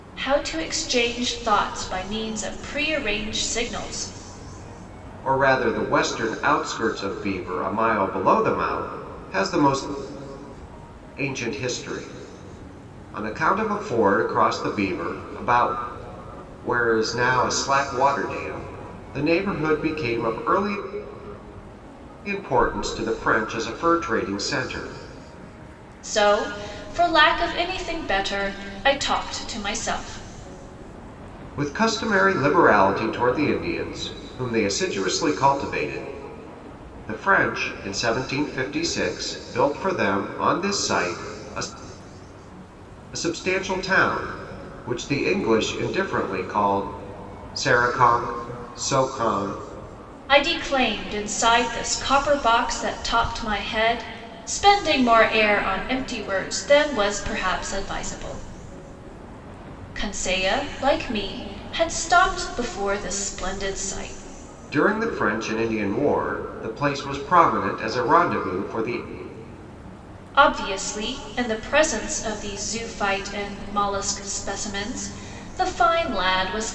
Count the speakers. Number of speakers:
2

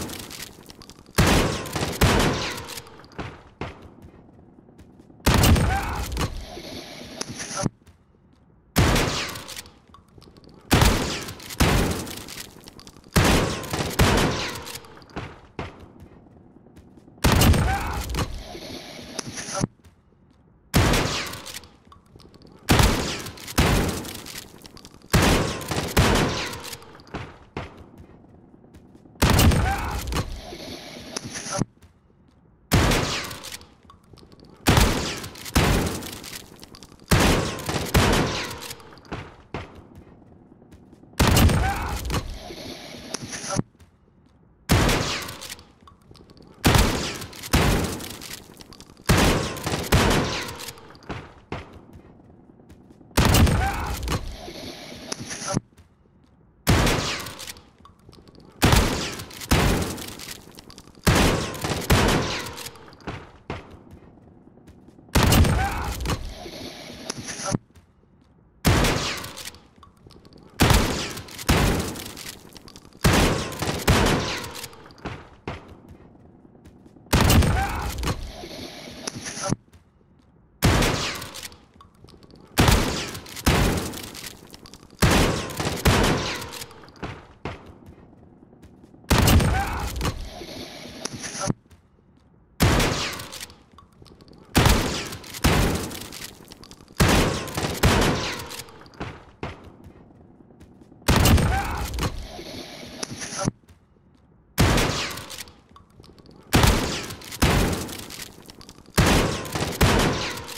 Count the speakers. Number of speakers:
0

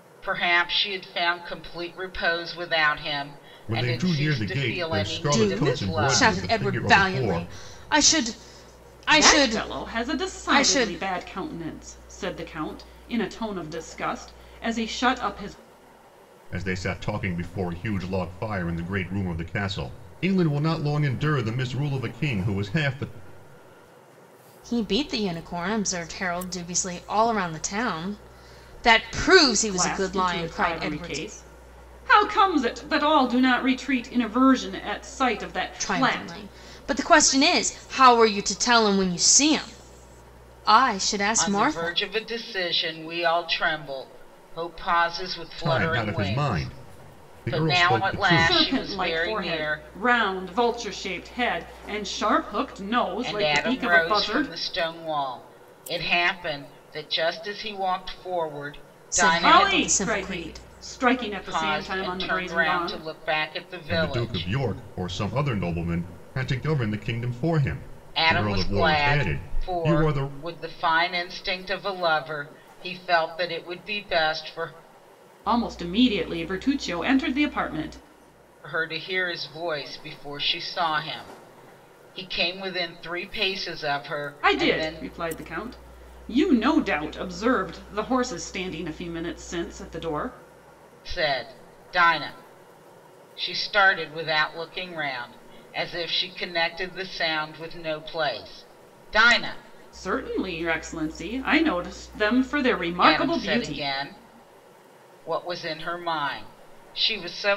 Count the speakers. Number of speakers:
4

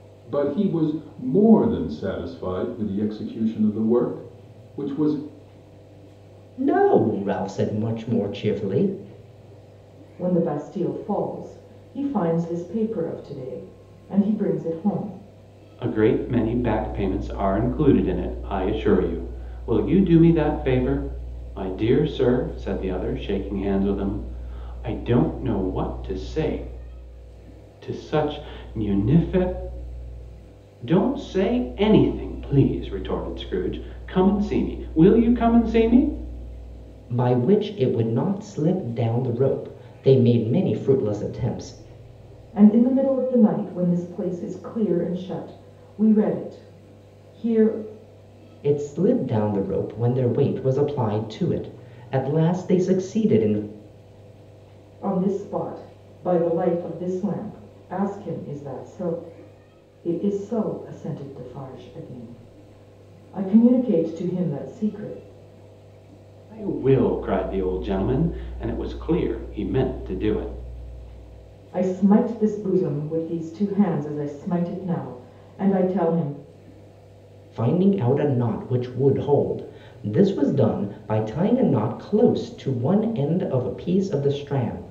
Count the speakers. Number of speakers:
4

